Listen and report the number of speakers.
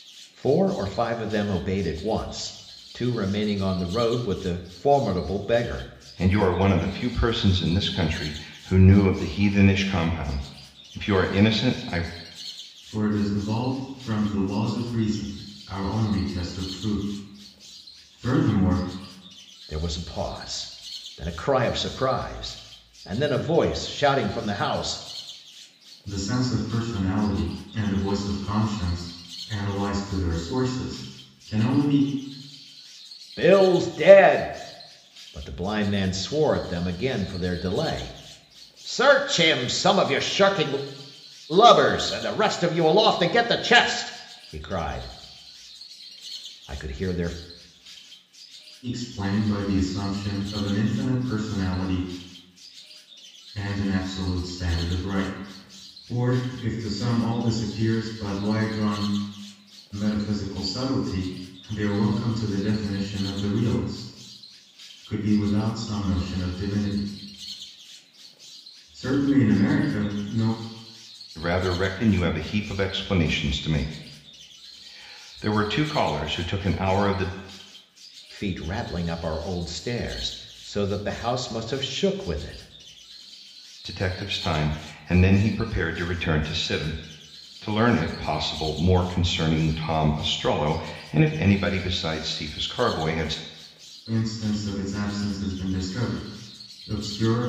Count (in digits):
3